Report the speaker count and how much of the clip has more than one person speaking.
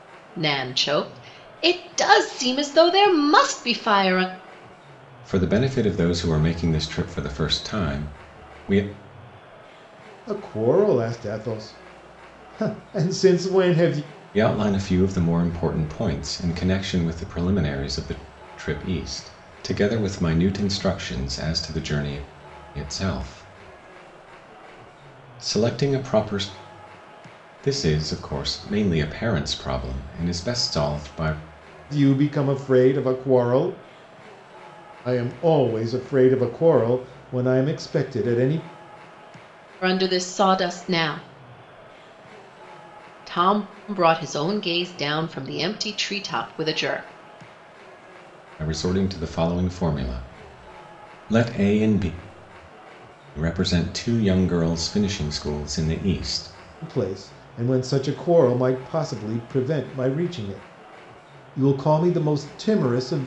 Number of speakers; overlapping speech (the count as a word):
three, no overlap